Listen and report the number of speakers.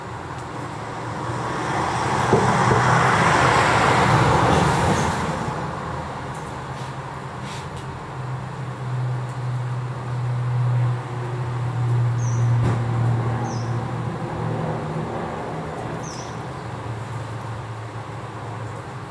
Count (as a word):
zero